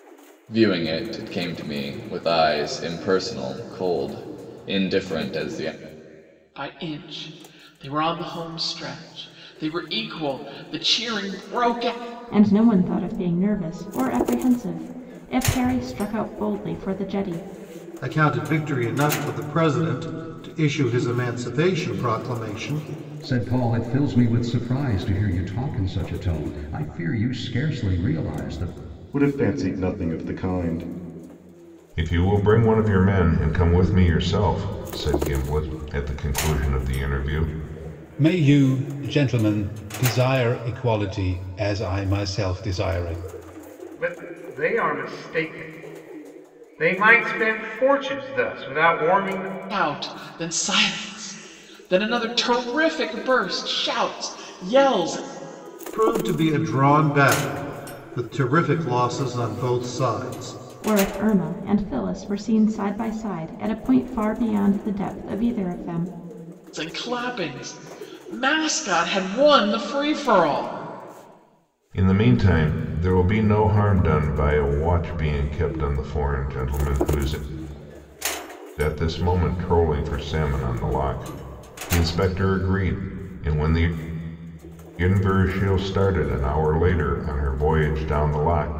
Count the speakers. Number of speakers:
9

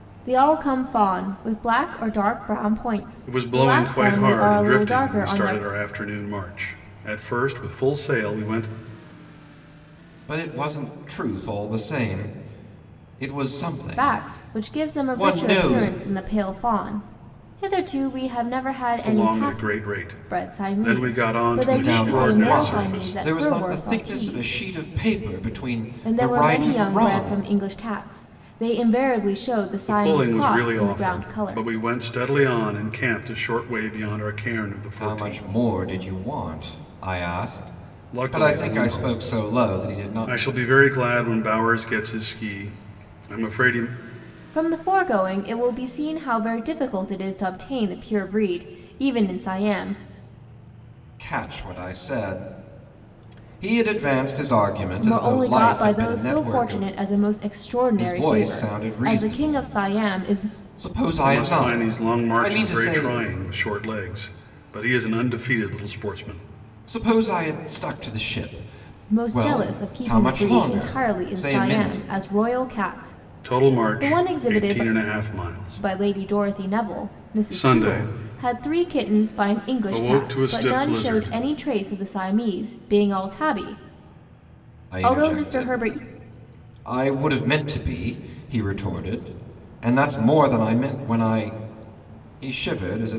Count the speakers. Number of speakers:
3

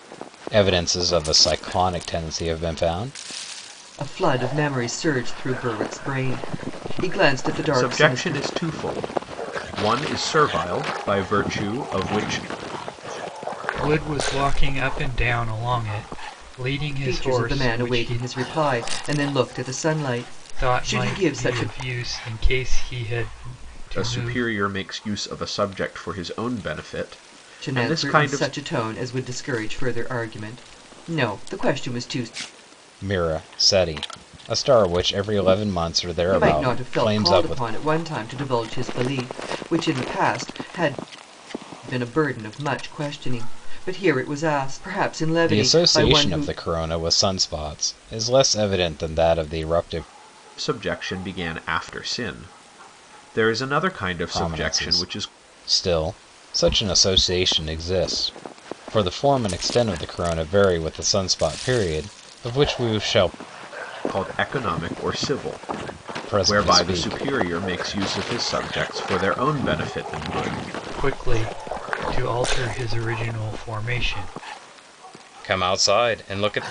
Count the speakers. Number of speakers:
4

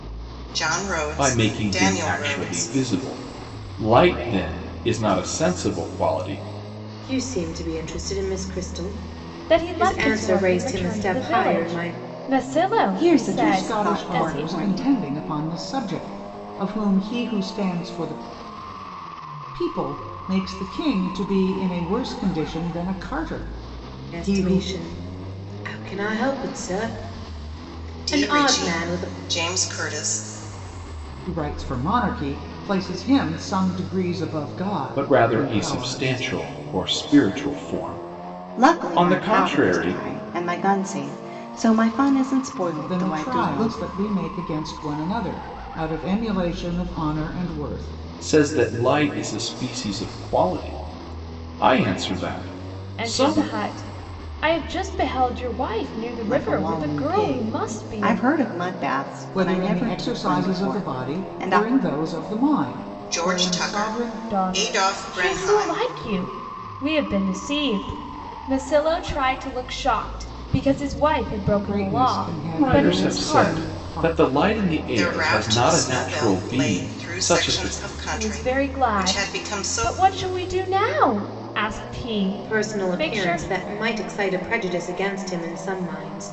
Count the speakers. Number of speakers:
6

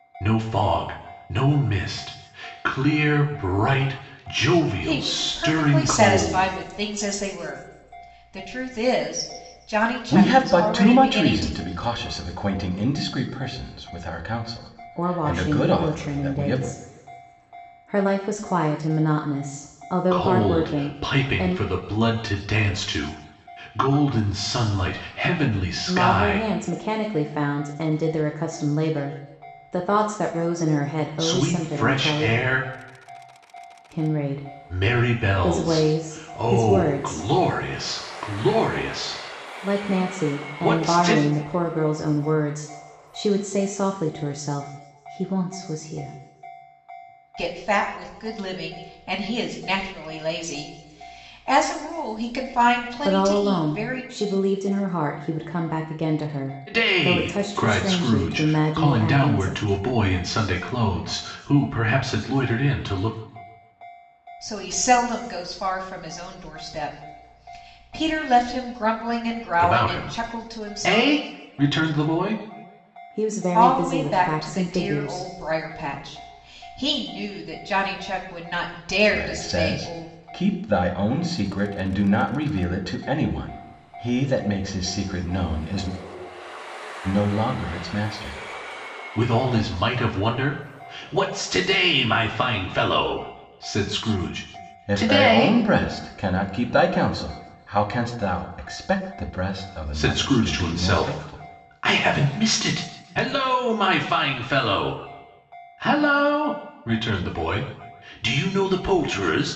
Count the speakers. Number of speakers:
4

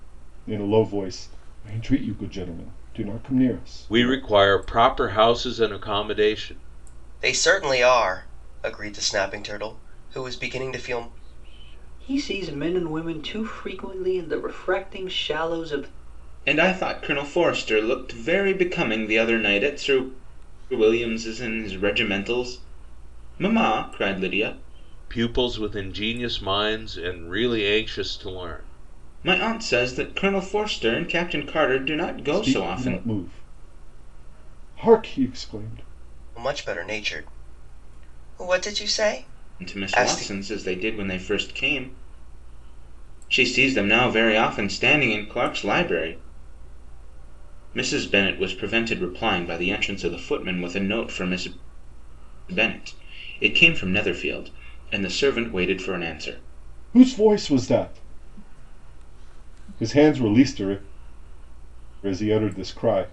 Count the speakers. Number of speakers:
5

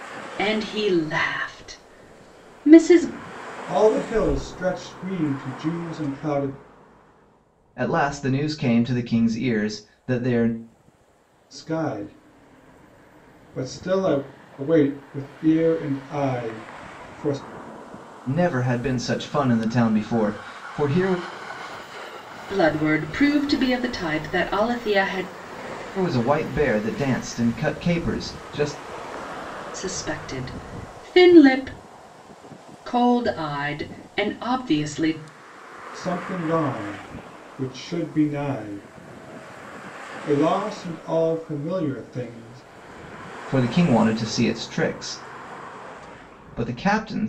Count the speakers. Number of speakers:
3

